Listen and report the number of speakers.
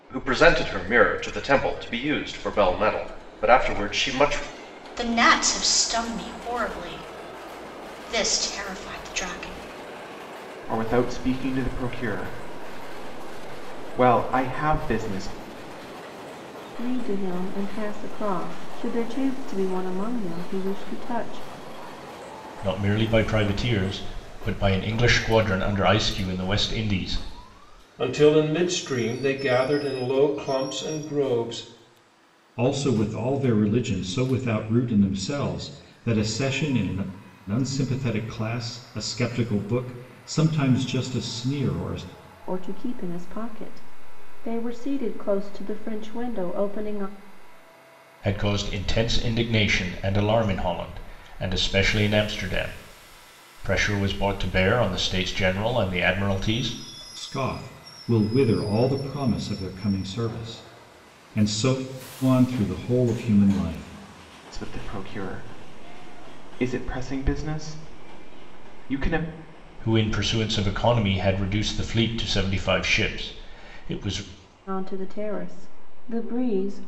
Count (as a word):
seven